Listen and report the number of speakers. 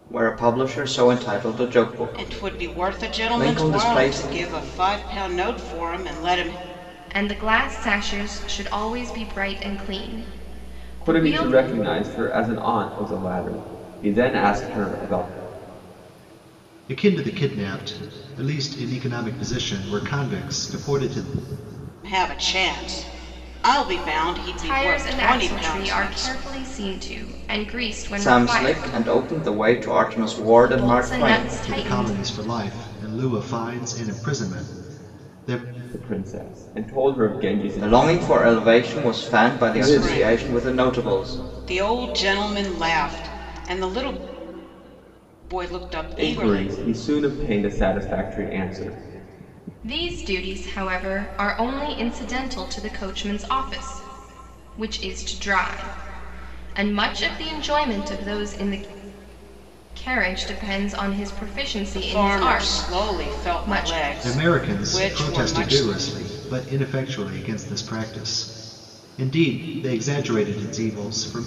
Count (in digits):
5